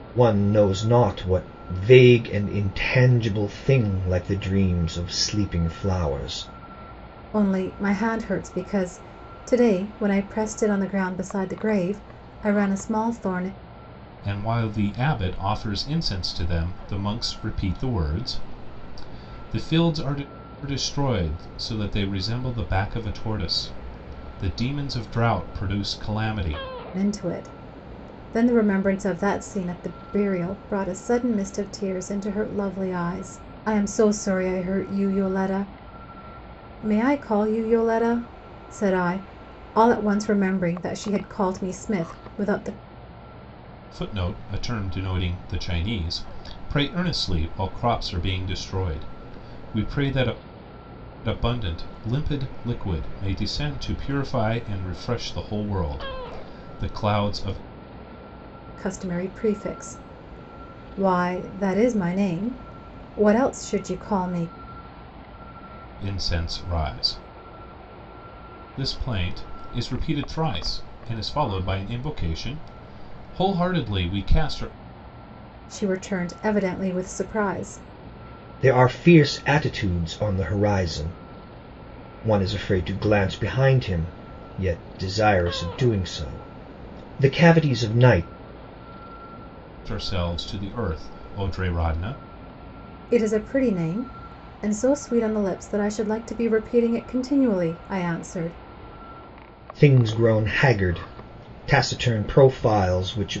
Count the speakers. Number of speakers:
three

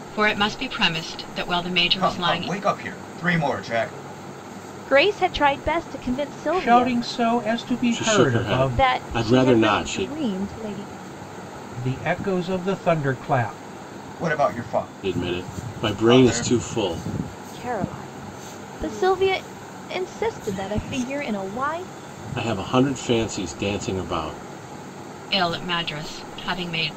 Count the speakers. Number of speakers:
five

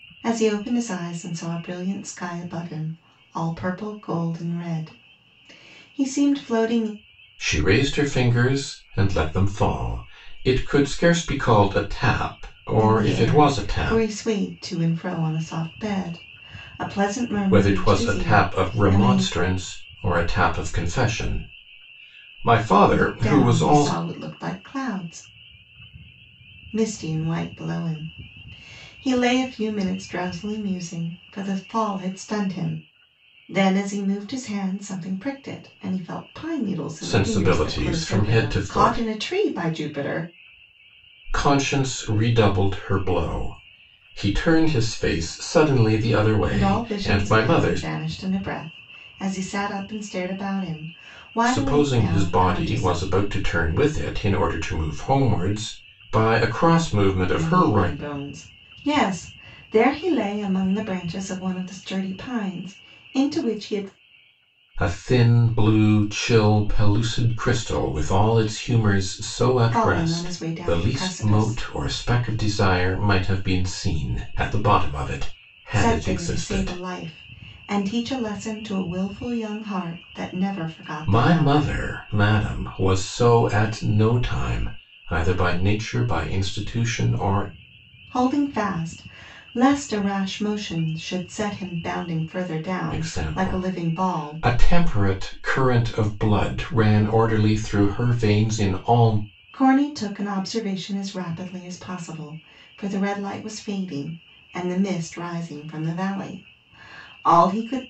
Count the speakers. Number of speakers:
two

